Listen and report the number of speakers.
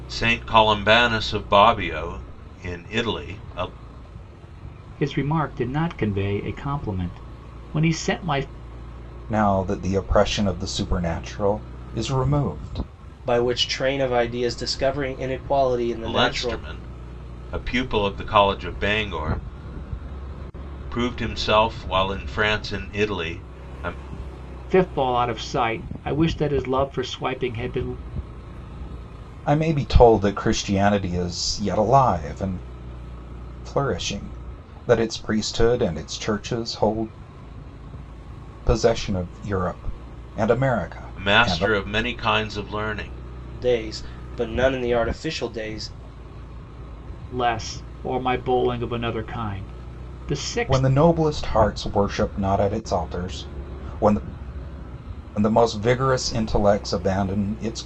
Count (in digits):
4